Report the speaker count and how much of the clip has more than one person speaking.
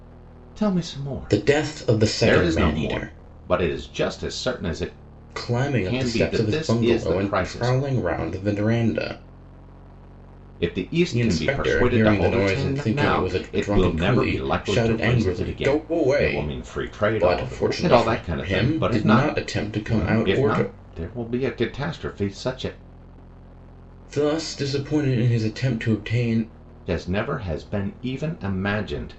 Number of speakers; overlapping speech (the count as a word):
two, about 45%